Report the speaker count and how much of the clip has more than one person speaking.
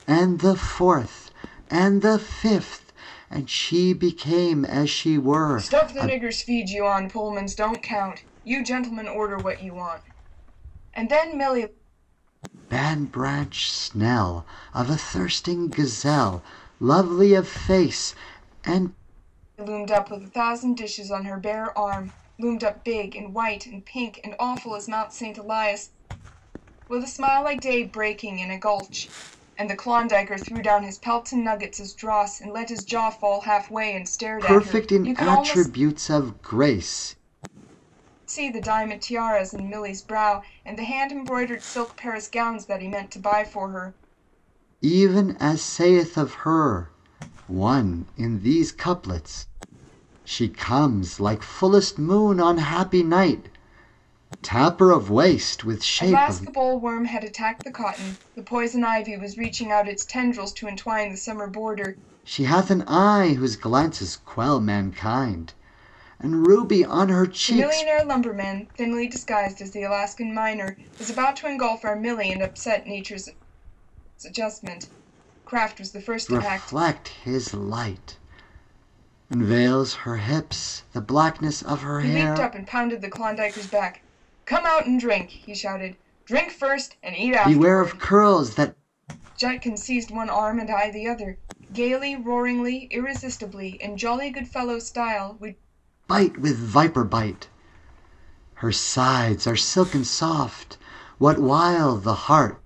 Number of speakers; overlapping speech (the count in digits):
2, about 5%